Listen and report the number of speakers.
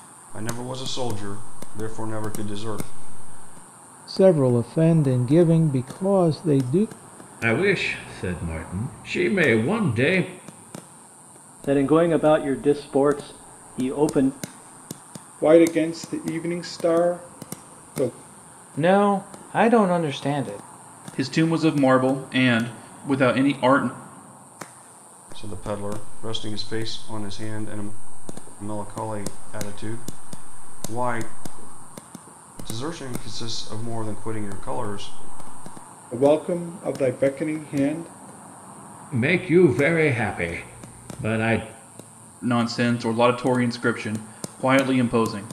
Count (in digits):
7